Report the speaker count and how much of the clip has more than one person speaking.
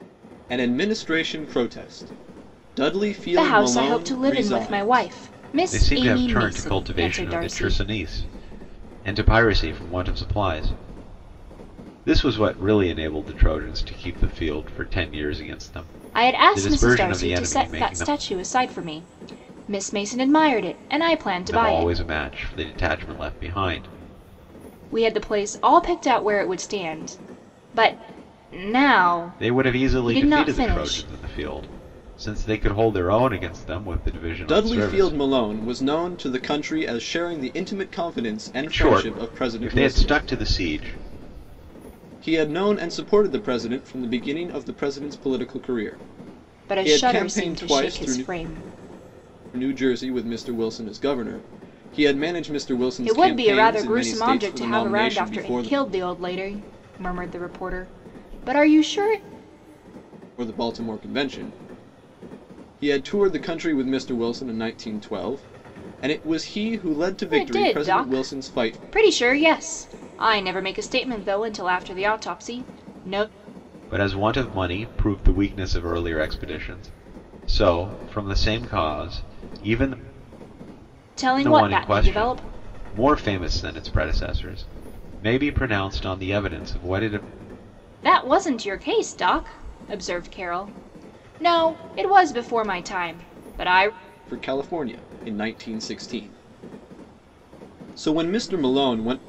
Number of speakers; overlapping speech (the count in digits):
3, about 18%